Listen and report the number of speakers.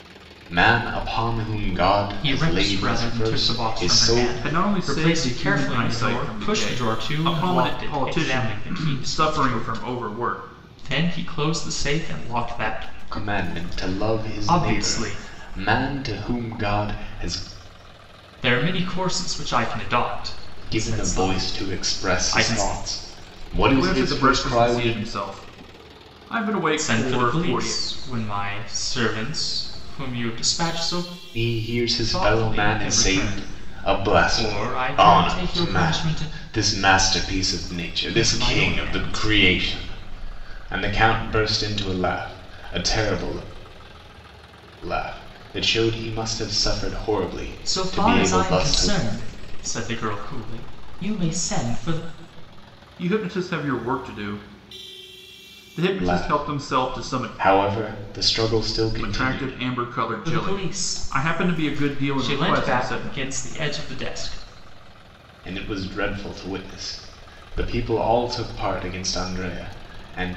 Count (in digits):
3